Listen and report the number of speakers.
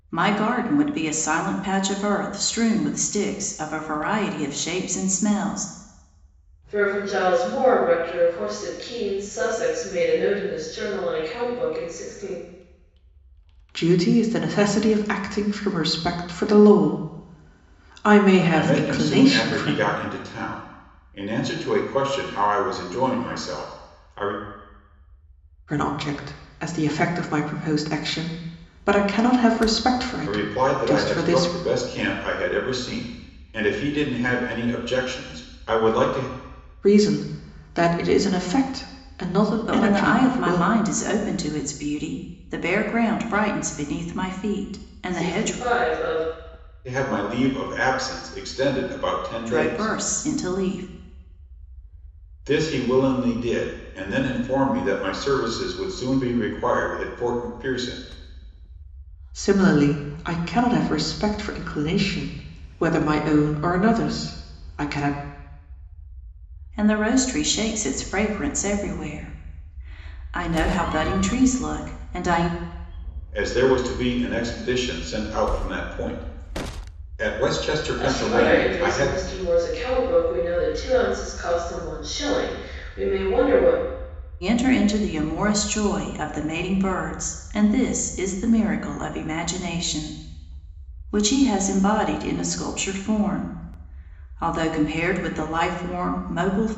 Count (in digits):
4